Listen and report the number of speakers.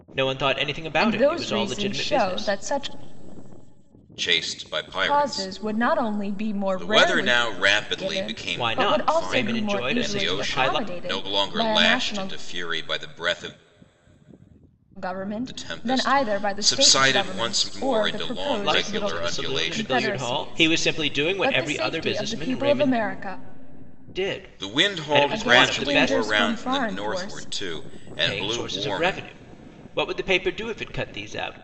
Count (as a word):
three